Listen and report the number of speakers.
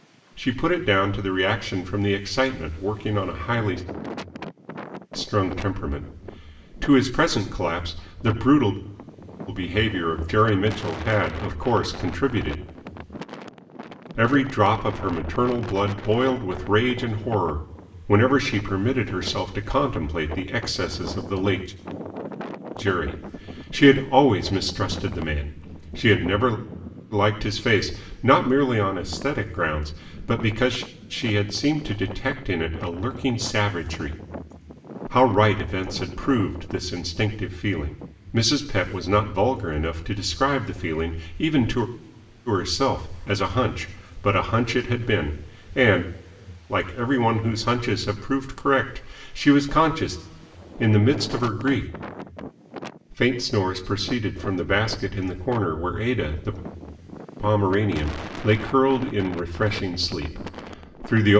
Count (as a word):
one